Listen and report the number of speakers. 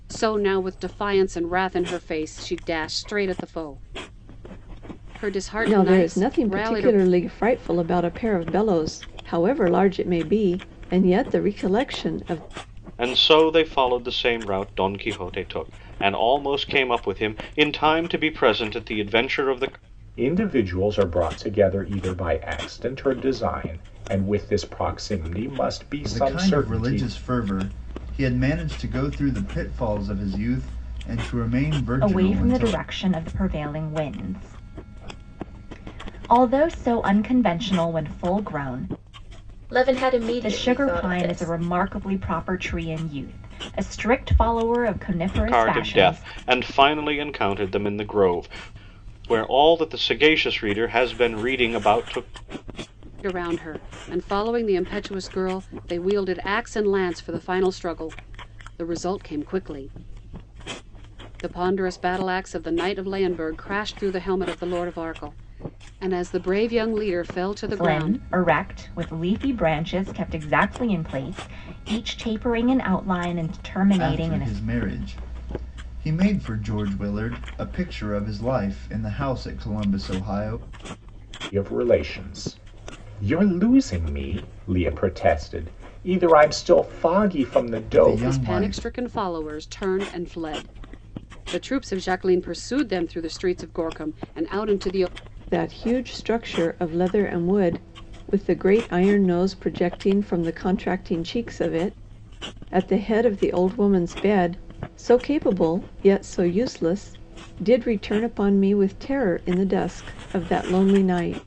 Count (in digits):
7